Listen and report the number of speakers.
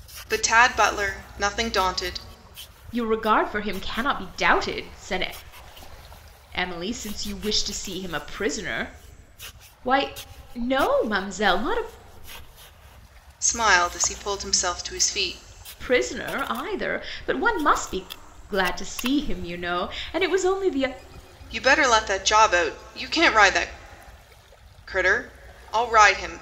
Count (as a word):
two